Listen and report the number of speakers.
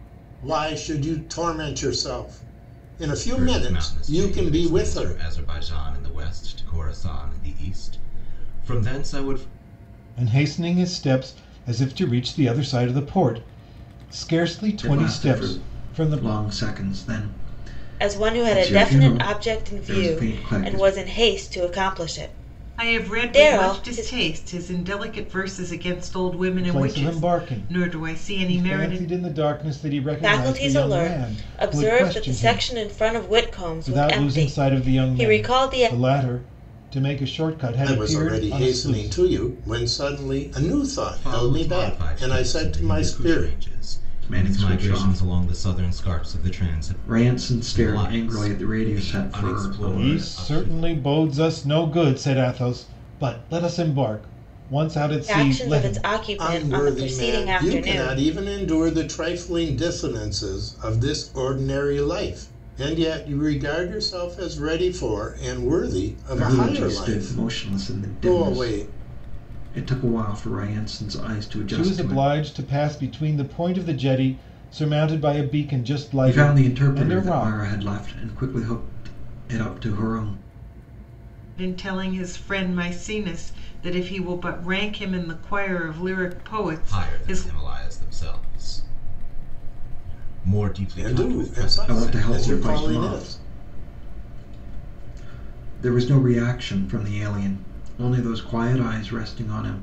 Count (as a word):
six